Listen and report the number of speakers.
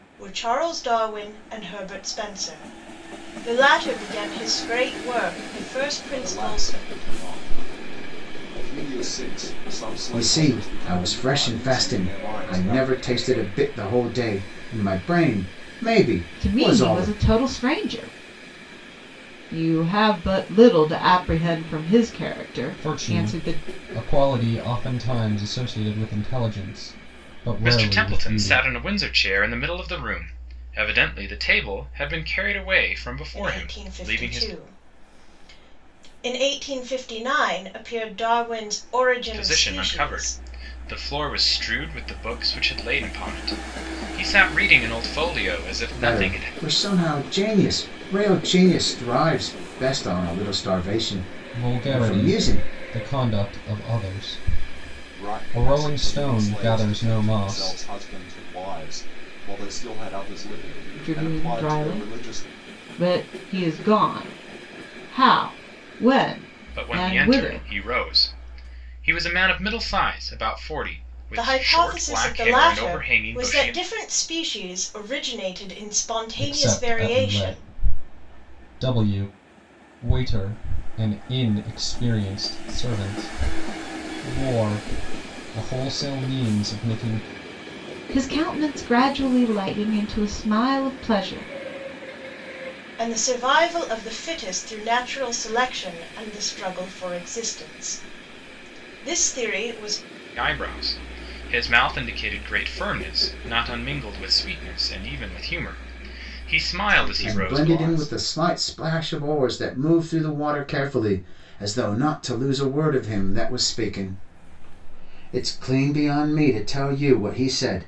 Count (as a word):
six